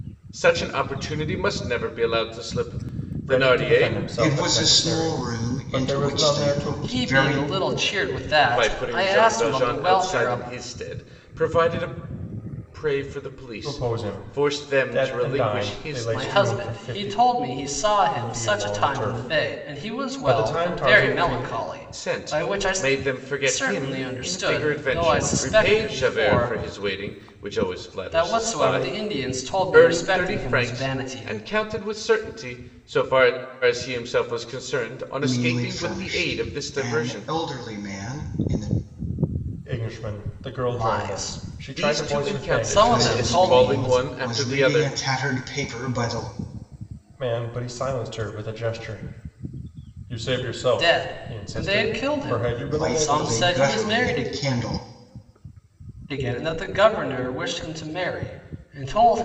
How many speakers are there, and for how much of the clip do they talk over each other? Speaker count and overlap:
4, about 49%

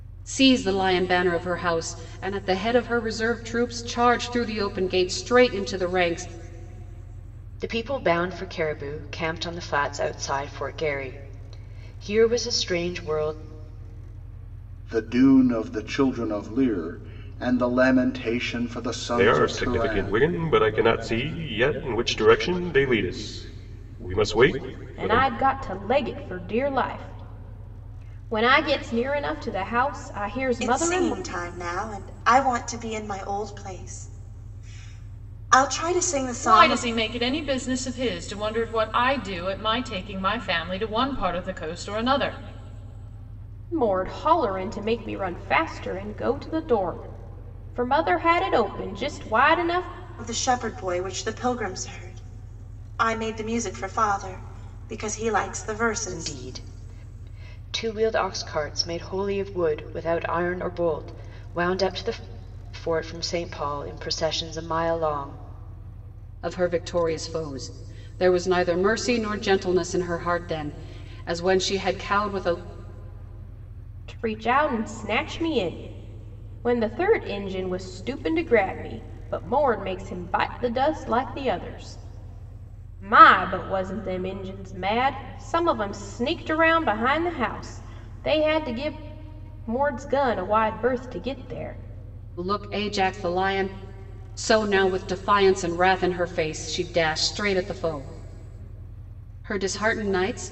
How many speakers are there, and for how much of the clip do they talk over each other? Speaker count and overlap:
7, about 3%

